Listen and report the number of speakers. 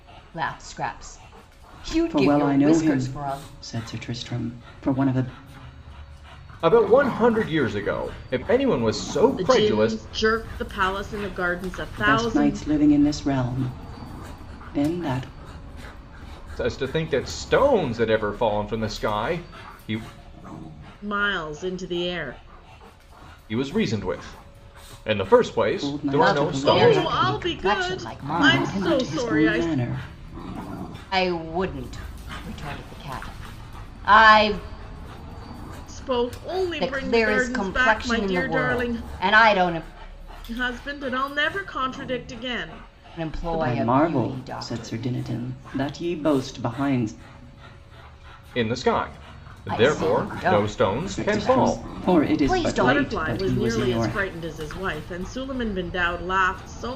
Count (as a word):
four